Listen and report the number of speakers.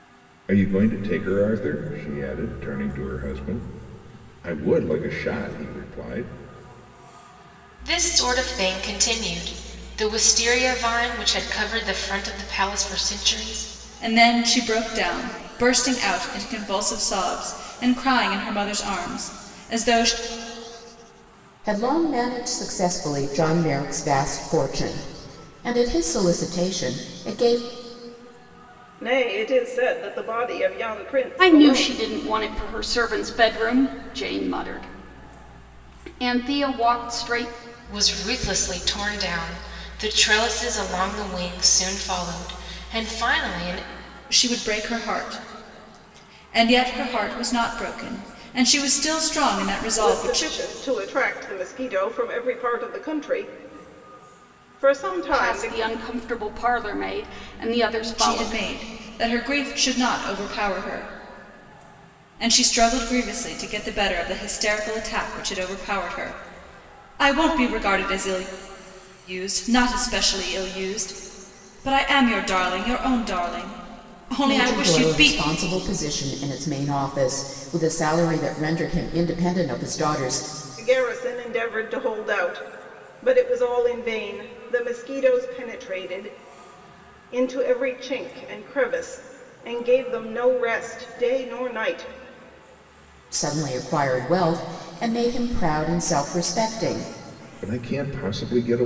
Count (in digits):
6